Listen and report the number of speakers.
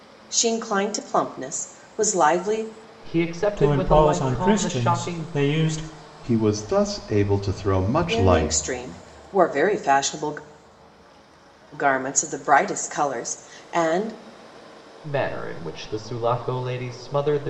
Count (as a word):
four